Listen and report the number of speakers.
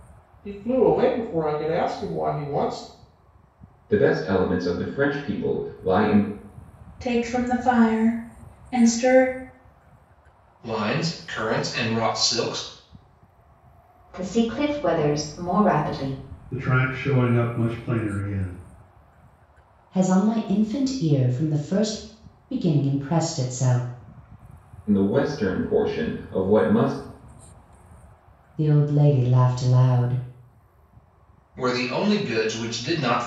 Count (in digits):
7